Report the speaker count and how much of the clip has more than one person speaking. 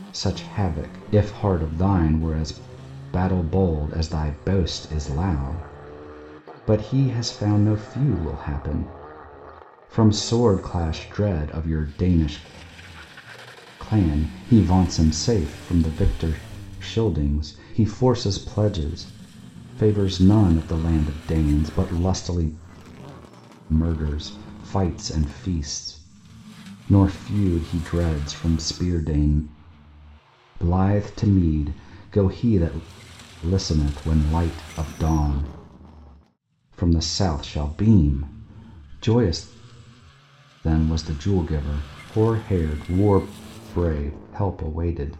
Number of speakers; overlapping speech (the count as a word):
one, no overlap